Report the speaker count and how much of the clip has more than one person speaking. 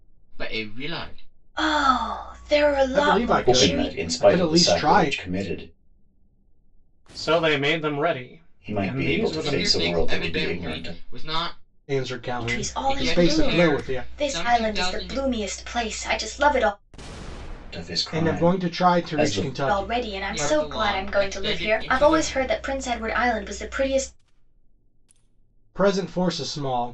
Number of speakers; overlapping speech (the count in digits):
5, about 42%